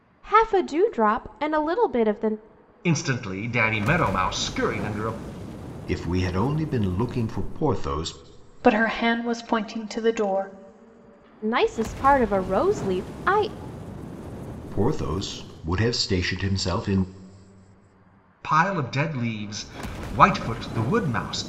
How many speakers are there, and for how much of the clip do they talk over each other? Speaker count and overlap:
four, no overlap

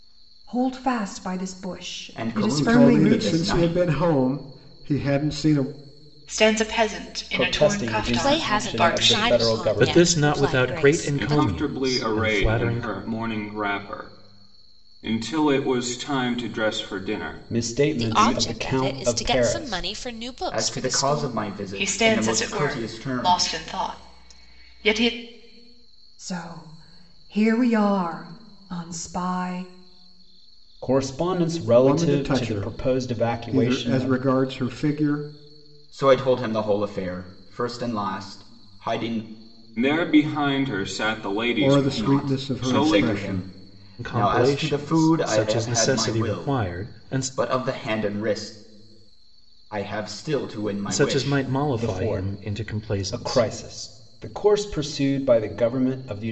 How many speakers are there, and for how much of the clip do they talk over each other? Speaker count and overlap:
eight, about 40%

